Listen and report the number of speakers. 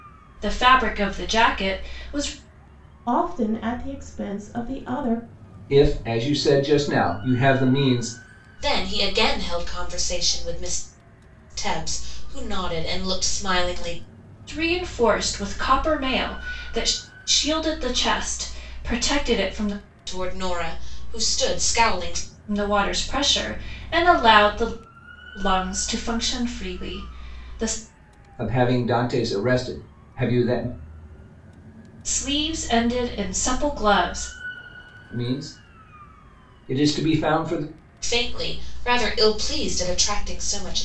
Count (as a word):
four